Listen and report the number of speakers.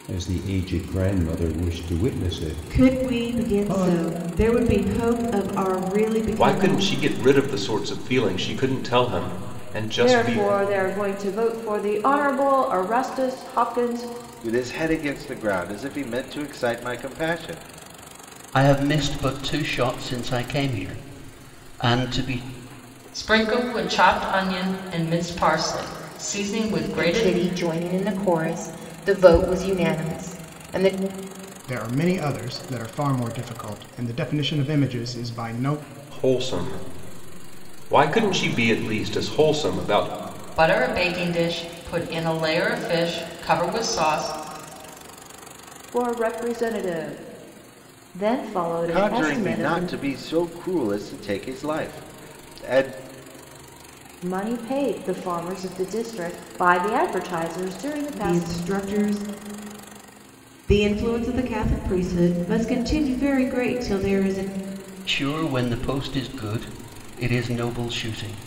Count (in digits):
9